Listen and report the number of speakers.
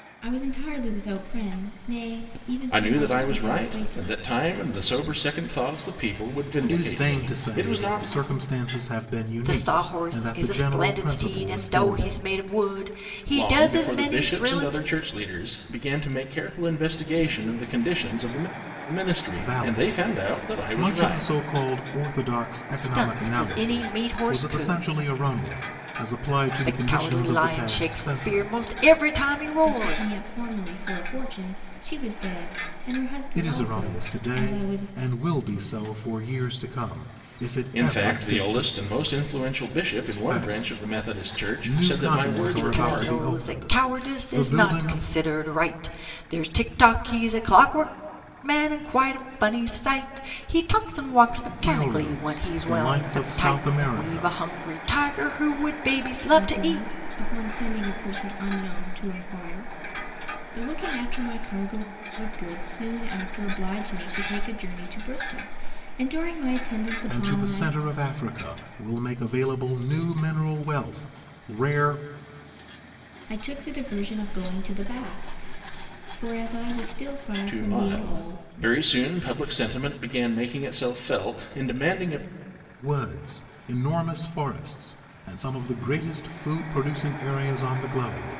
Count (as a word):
four